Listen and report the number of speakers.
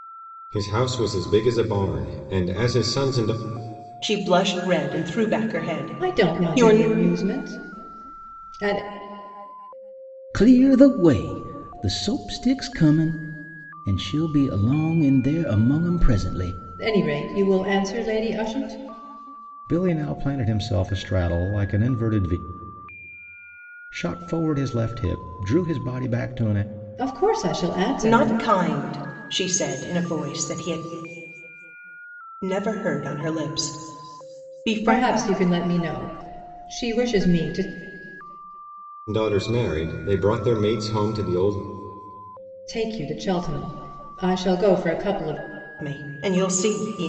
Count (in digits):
4